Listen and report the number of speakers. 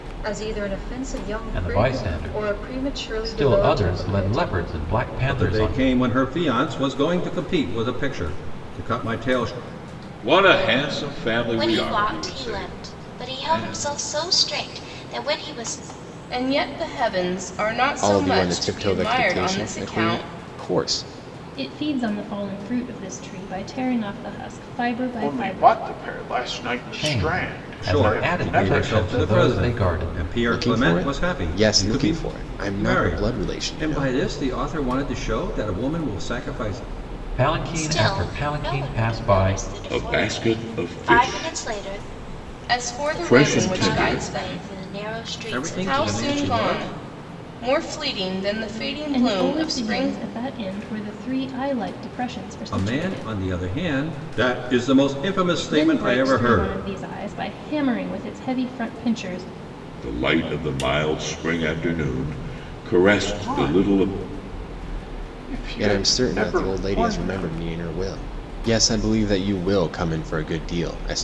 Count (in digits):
9